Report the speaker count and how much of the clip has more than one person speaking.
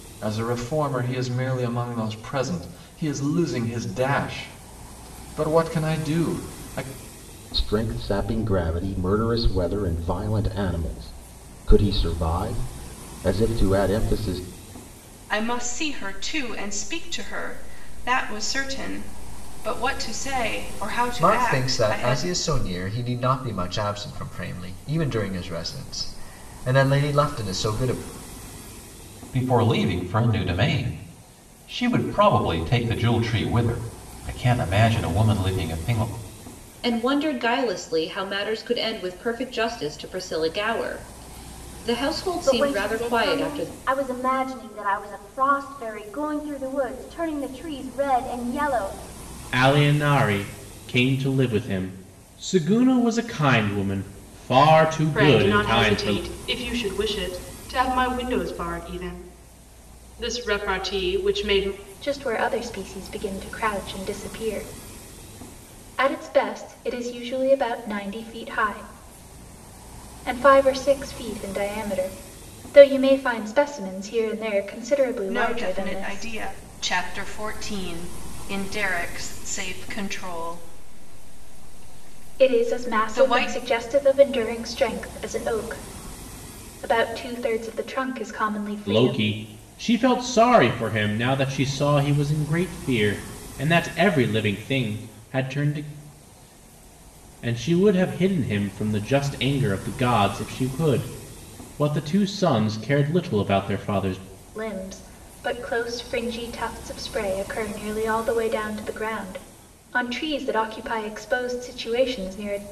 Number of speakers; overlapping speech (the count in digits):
10, about 6%